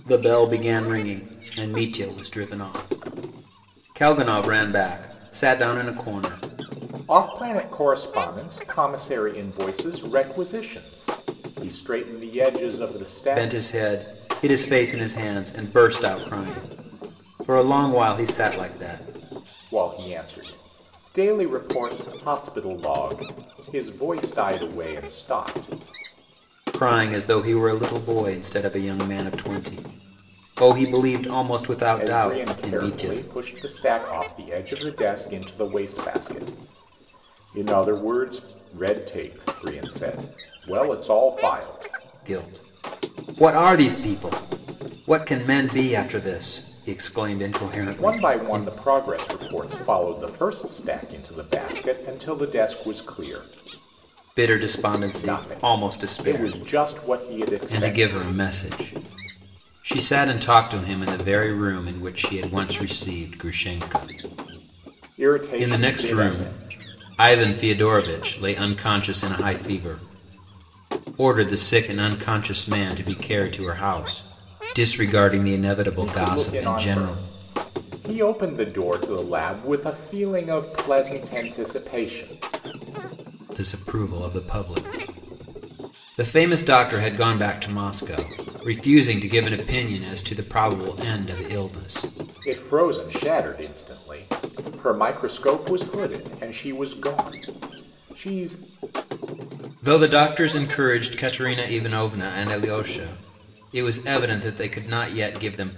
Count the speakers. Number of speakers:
2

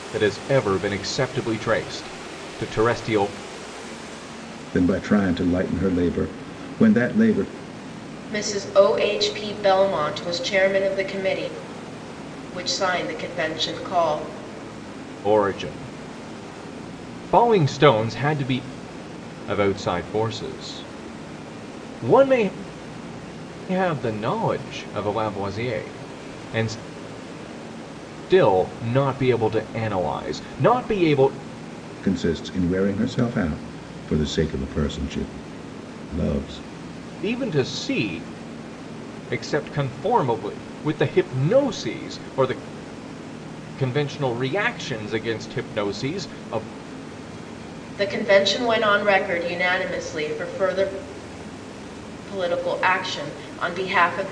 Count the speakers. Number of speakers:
3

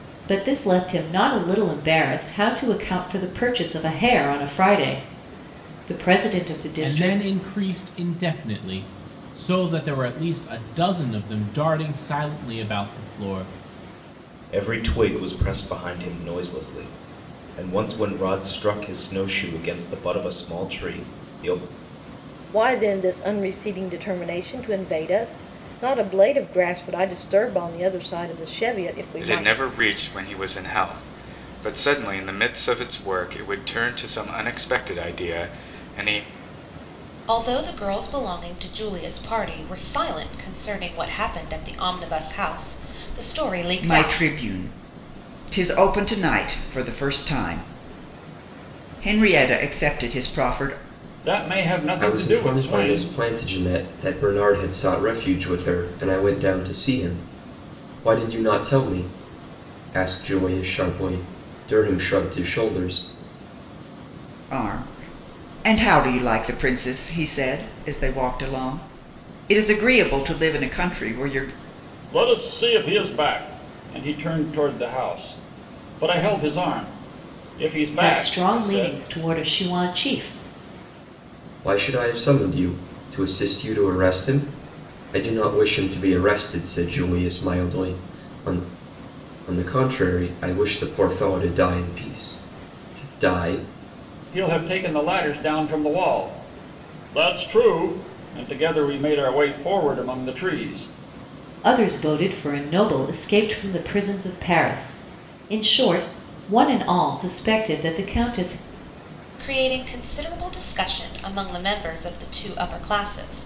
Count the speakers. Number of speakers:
9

